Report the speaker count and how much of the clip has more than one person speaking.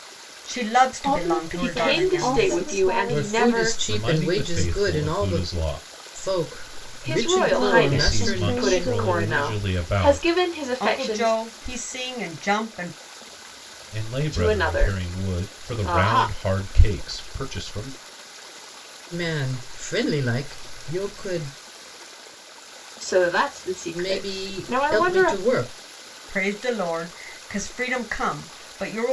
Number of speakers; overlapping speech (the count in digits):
5, about 41%